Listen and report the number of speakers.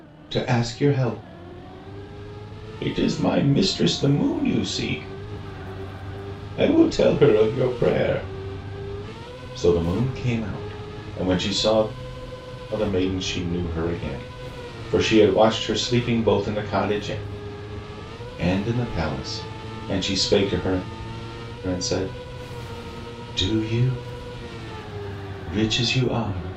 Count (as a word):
one